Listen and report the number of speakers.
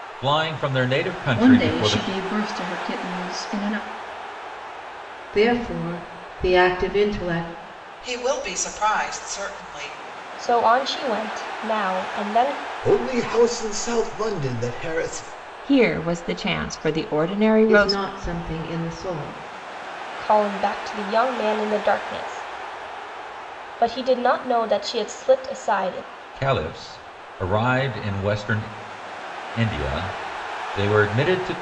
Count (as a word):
seven